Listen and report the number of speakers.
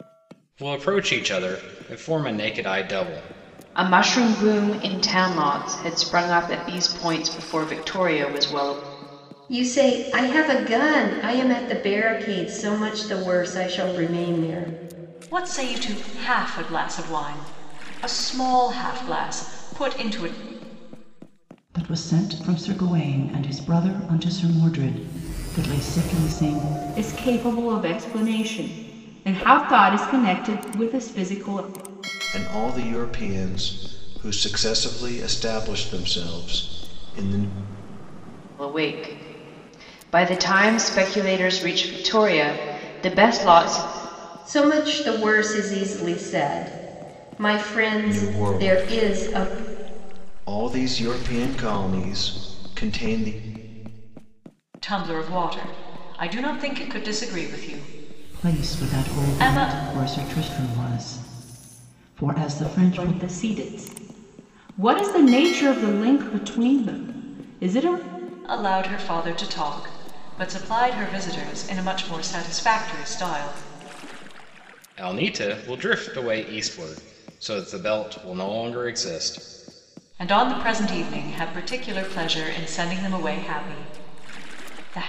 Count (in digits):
7